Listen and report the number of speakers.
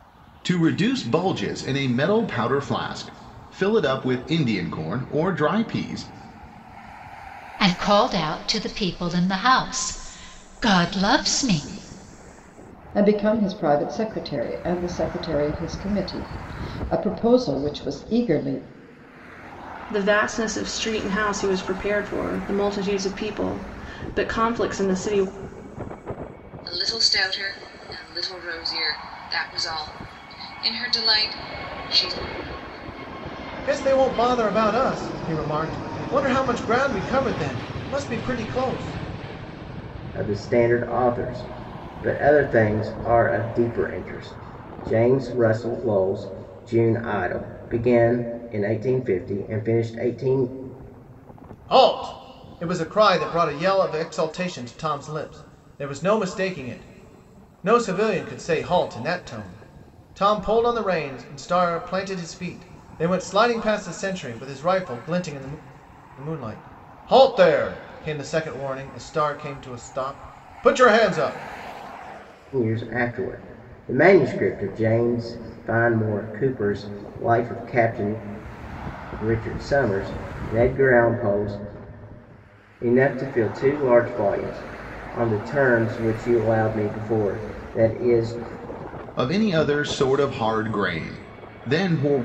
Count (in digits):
7